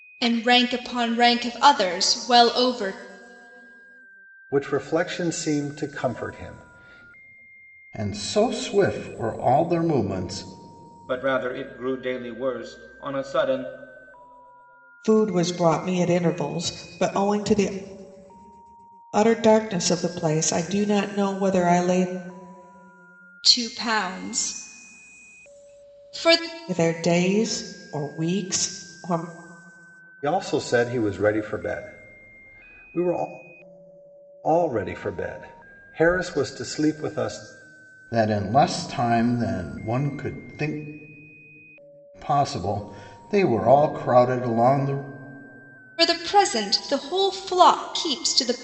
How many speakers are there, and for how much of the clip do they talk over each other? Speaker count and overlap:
five, no overlap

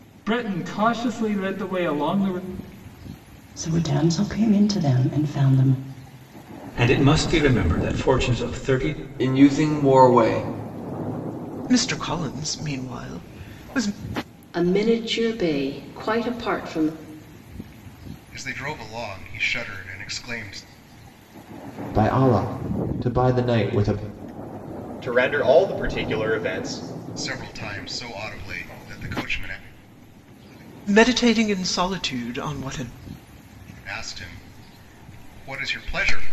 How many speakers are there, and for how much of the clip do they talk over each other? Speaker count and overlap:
nine, no overlap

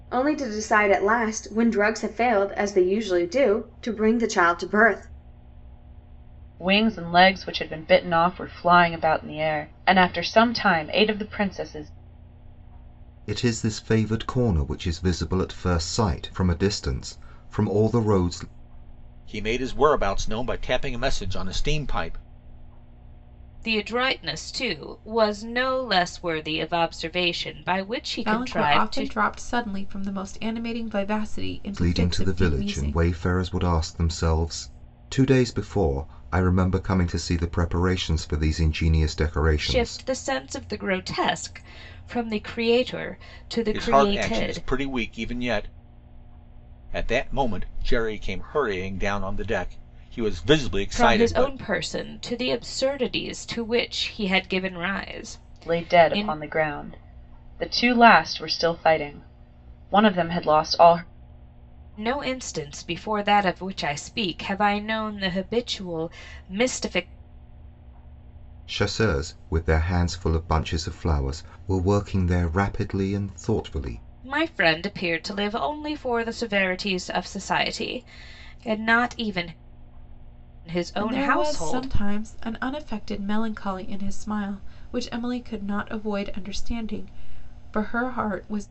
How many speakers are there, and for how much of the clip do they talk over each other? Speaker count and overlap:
six, about 7%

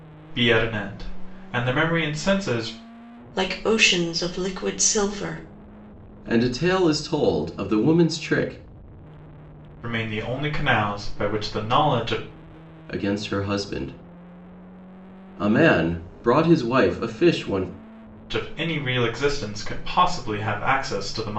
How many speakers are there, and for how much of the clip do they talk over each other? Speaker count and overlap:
three, no overlap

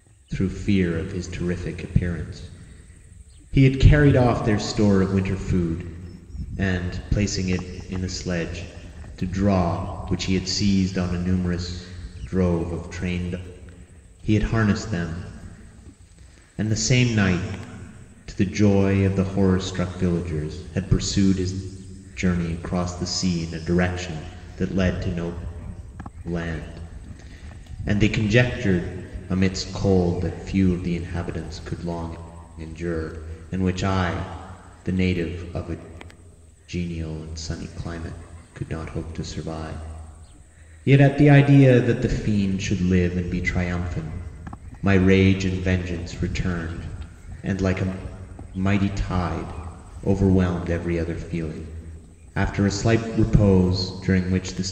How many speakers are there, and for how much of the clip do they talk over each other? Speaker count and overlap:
one, no overlap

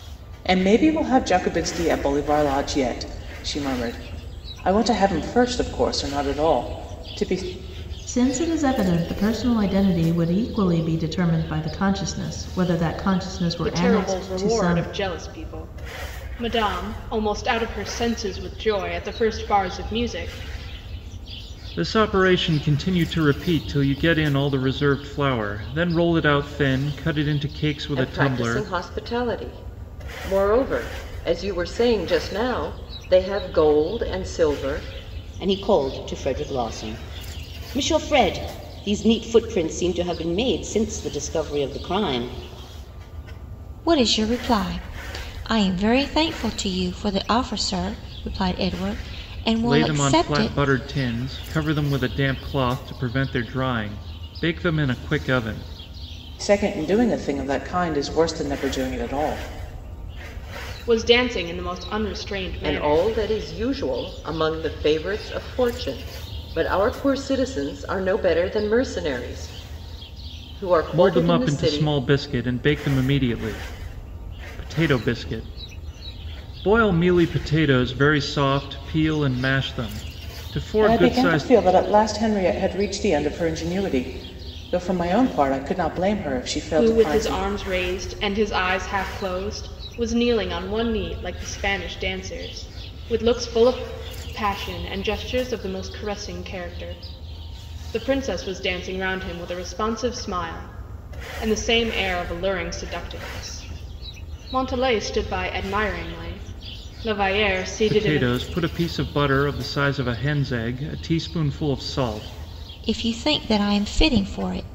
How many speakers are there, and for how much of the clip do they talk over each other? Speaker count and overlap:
seven, about 6%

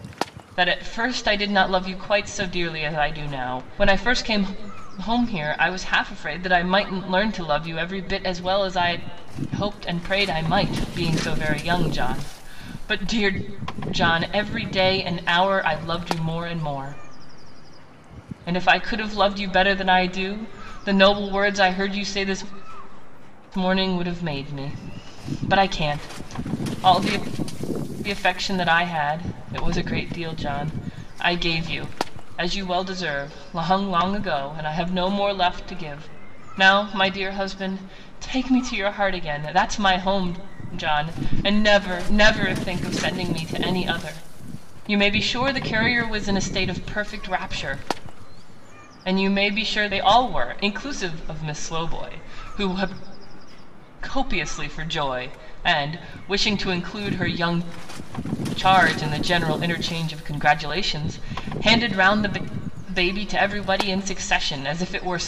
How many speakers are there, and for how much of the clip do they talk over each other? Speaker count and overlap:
one, no overlap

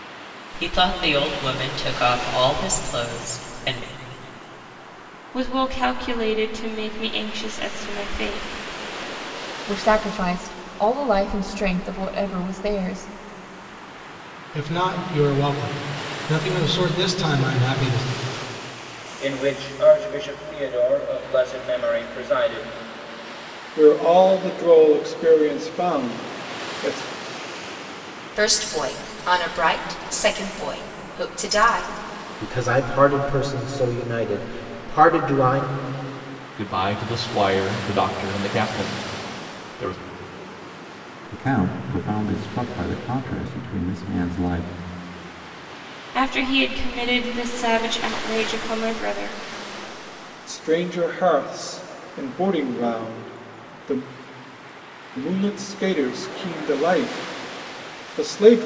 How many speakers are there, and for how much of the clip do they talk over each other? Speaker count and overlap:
ten, no overlap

